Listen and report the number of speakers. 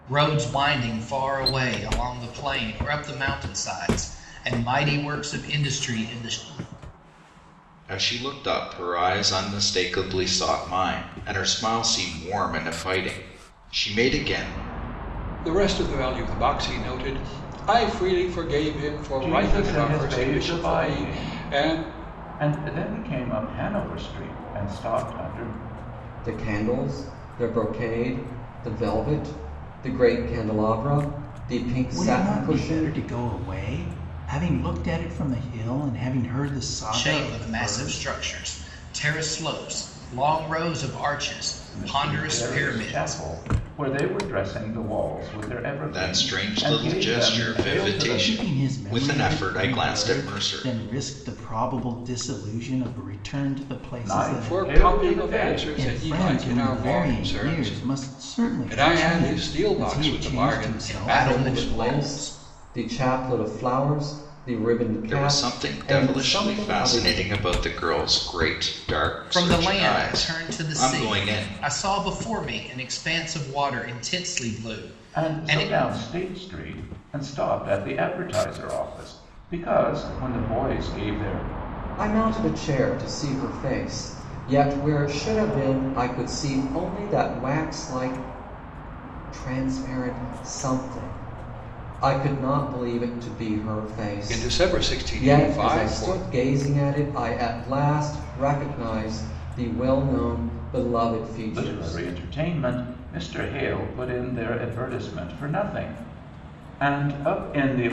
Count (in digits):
6